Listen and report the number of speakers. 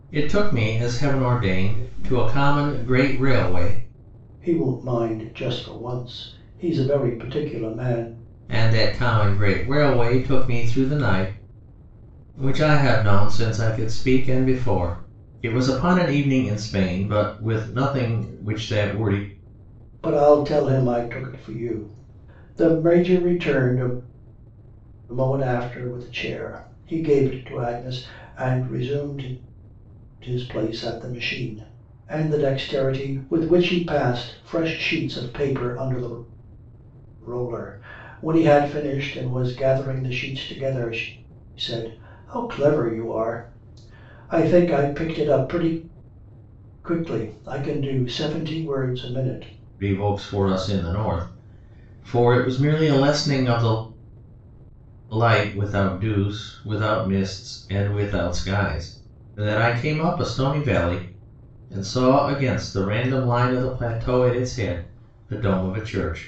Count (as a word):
two